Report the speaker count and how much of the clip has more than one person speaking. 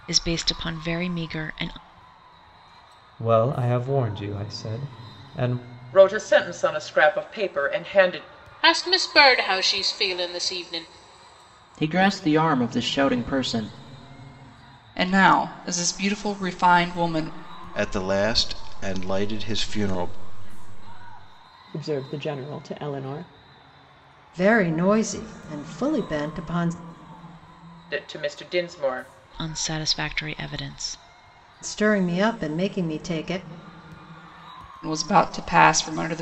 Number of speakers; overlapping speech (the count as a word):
nine, no overlap